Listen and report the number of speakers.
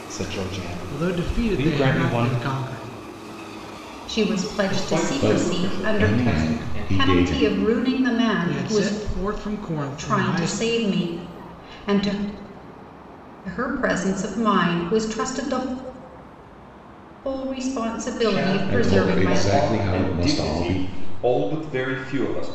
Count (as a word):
five